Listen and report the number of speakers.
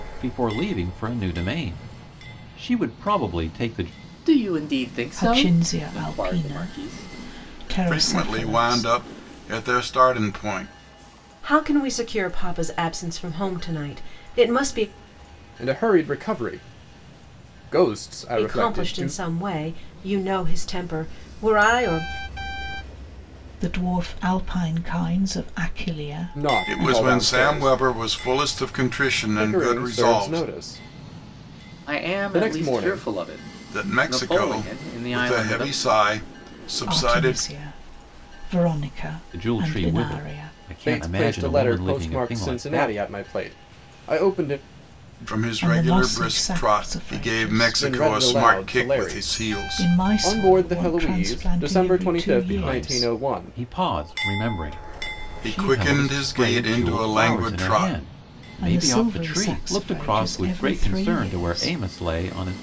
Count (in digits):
6